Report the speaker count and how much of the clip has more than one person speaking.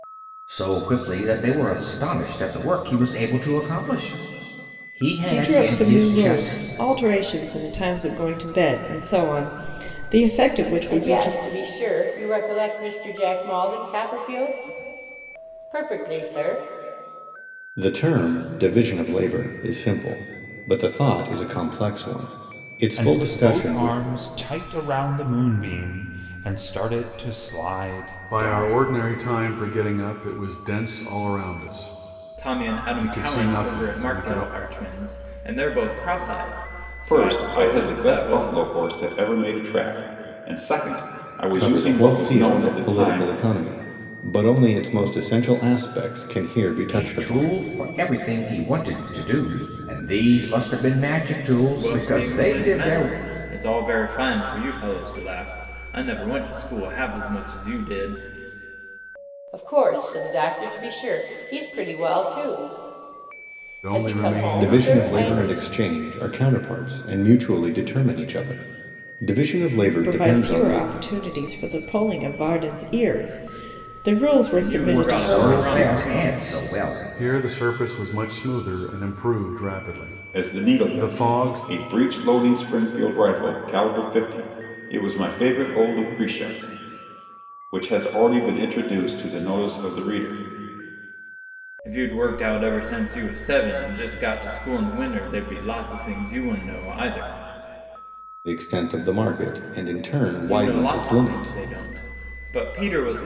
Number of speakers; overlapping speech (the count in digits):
8, about 19%